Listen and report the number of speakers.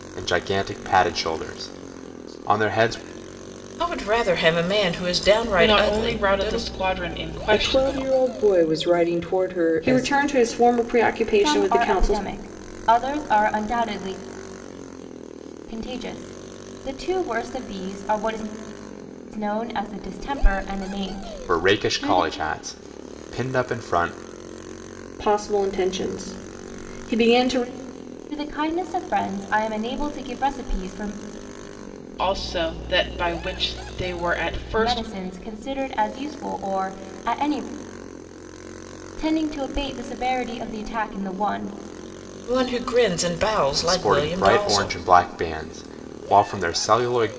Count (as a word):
six